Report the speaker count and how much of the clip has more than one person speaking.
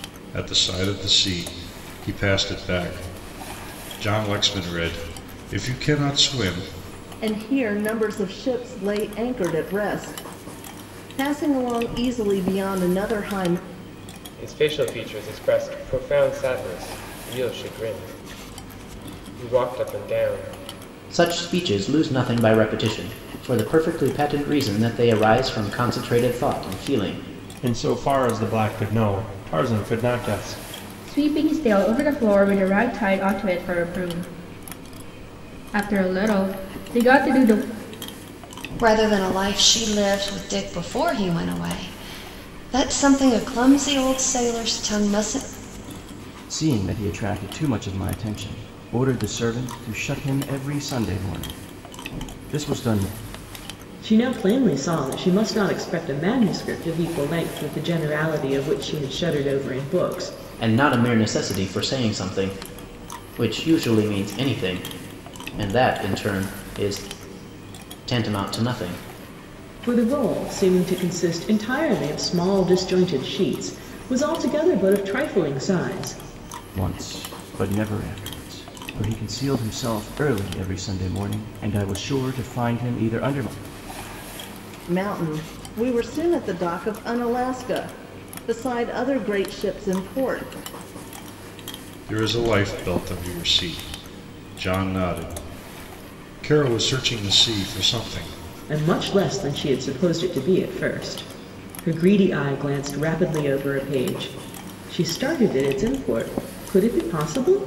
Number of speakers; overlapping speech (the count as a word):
nine, no overlap